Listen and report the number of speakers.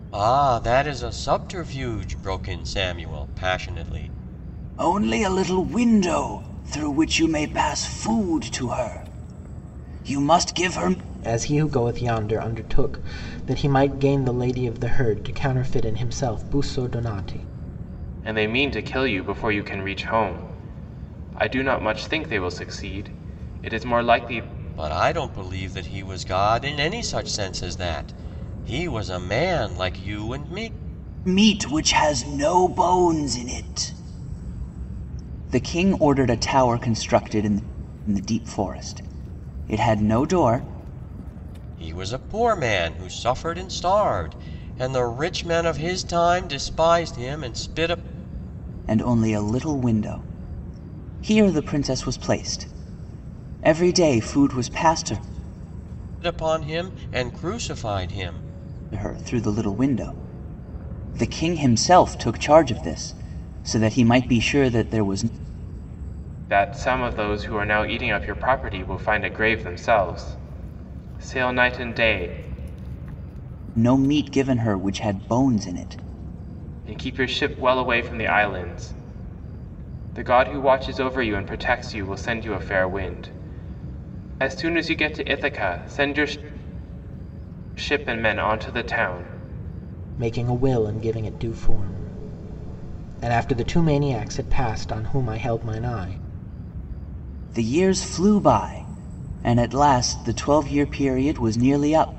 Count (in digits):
4